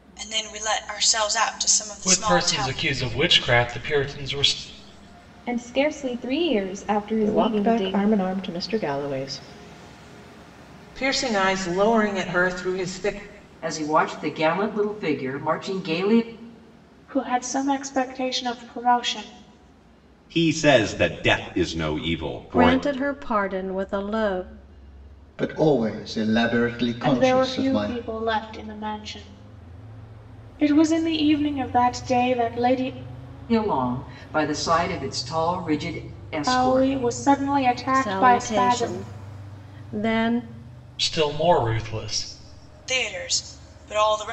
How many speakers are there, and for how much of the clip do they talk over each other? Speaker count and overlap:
10, about 11%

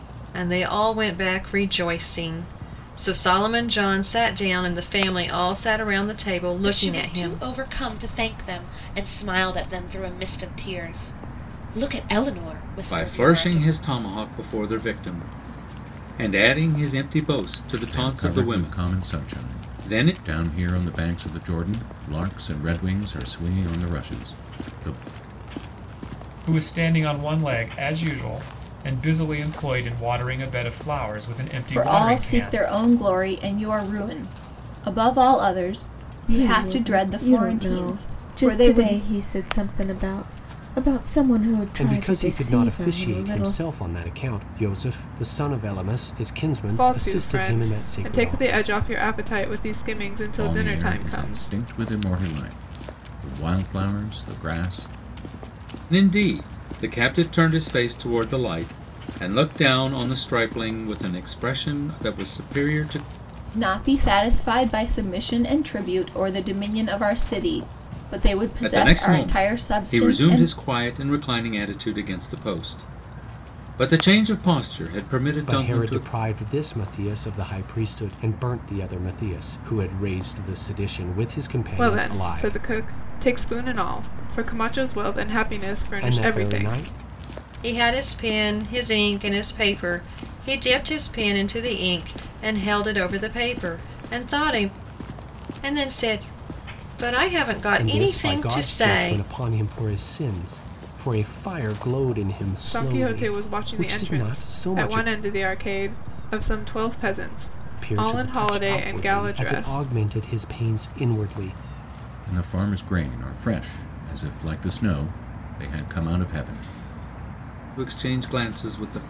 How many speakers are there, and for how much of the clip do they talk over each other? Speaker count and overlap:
9, about 20%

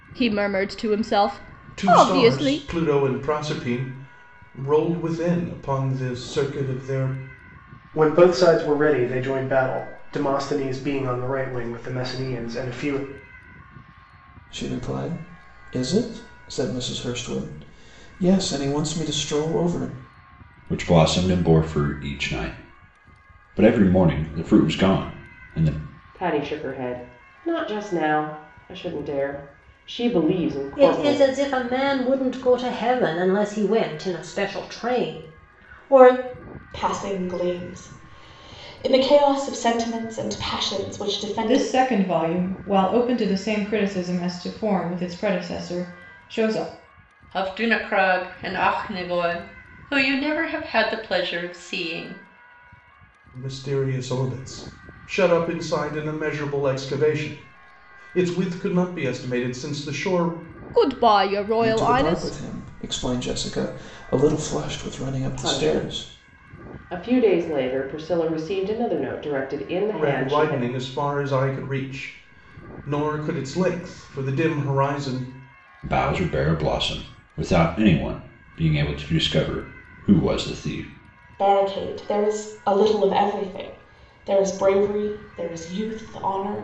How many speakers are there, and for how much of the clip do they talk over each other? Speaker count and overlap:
10, about 5%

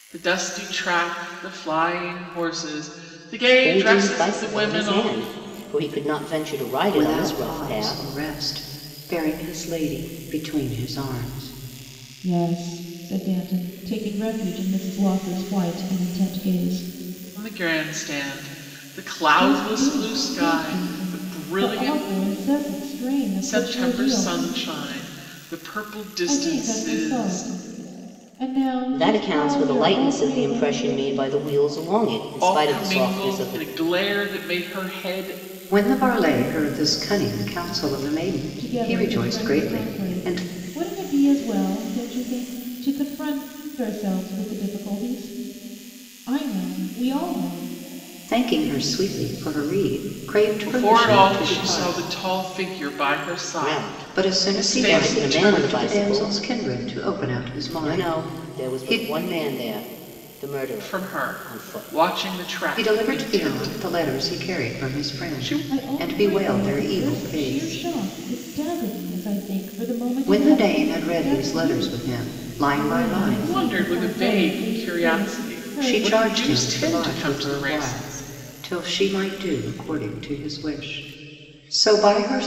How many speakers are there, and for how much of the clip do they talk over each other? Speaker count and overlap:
4, about 39%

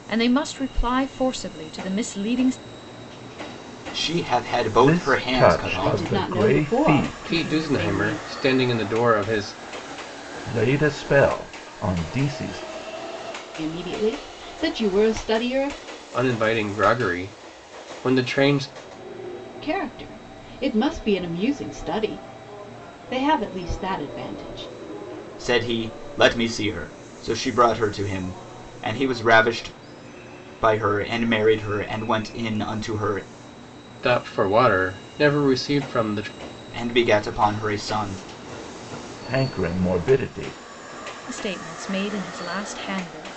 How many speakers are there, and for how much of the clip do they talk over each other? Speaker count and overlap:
5, about 8%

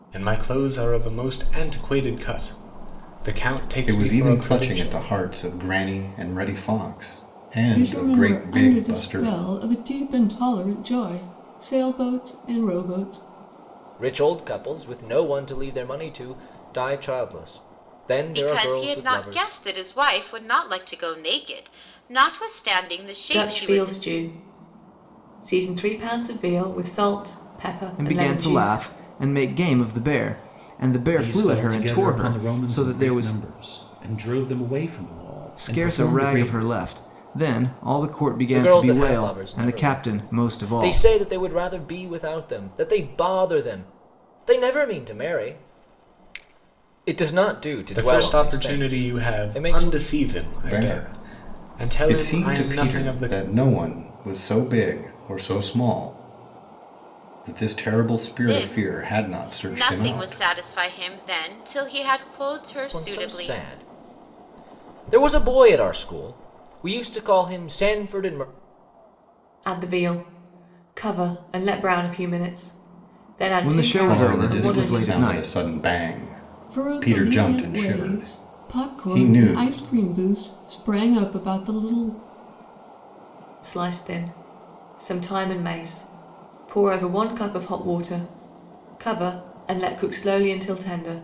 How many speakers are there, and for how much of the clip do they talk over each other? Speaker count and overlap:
8, about 26%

